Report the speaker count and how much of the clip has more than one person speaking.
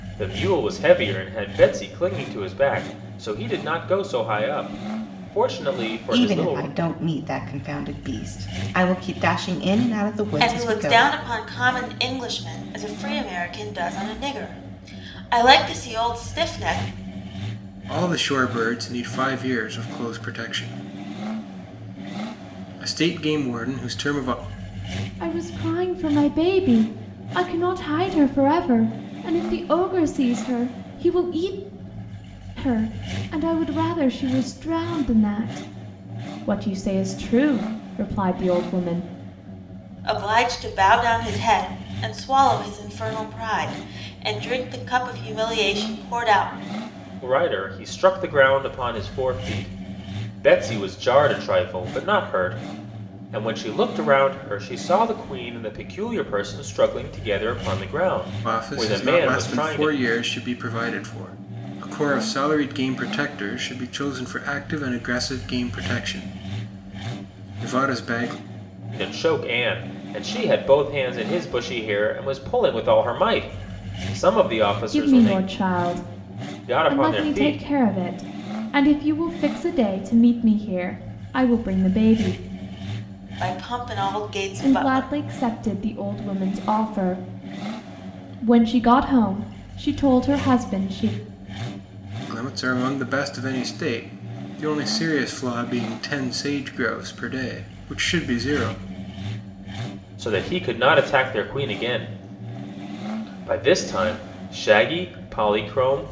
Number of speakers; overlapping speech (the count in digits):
5, about 4%